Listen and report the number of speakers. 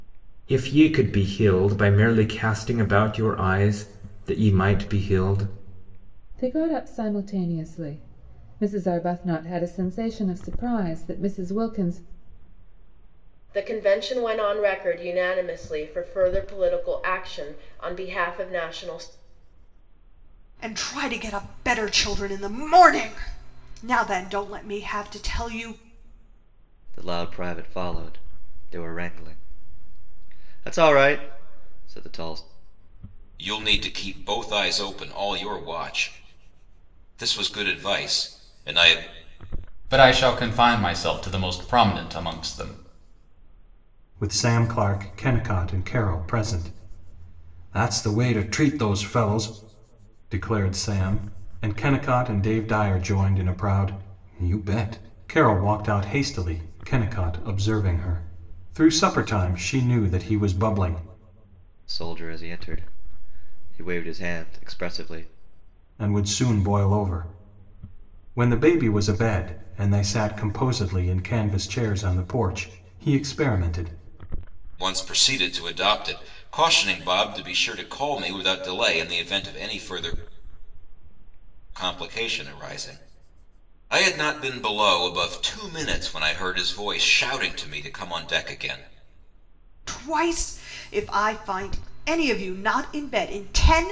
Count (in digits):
8